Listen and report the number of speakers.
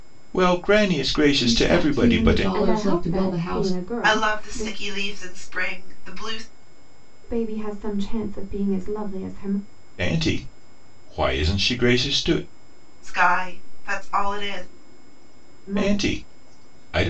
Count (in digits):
4